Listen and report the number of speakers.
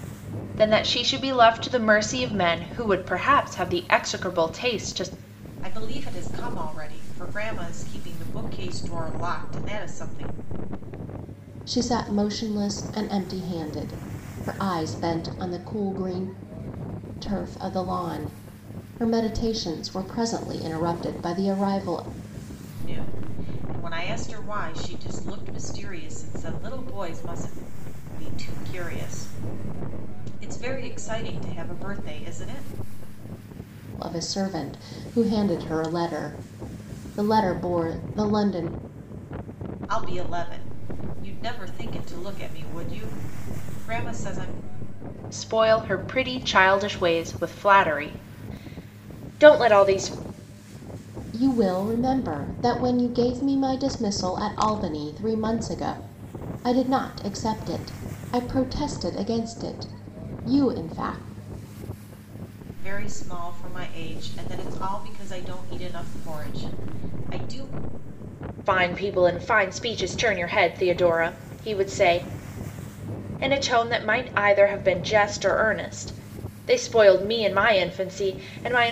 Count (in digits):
3